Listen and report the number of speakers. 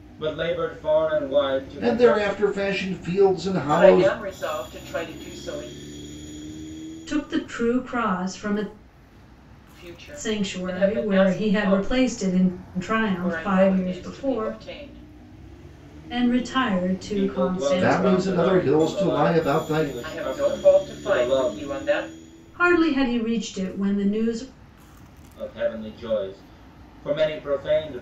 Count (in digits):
4